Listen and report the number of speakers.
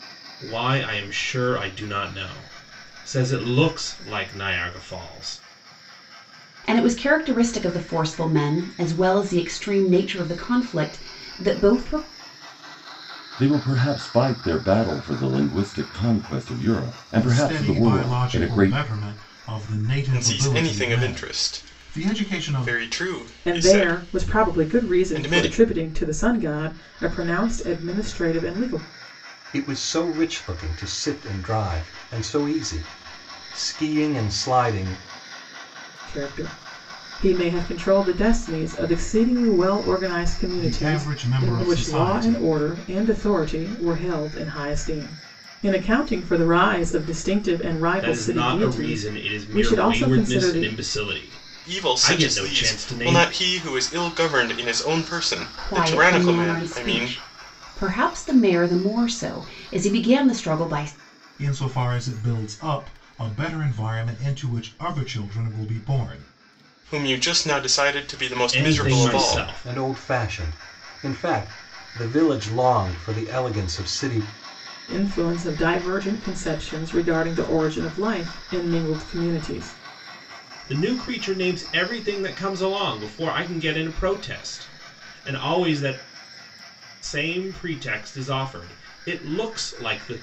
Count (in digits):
7